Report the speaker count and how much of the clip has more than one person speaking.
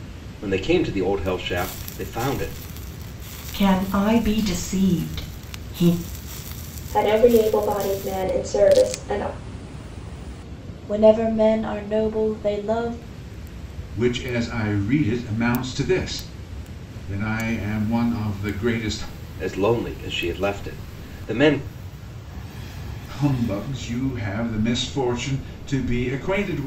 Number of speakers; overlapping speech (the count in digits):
5, no overlap